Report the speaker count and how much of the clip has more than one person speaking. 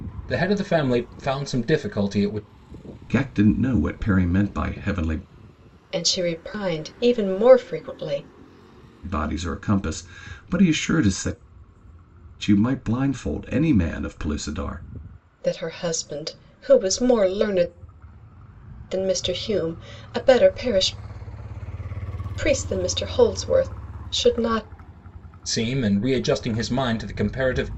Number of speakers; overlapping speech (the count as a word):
three, no overlap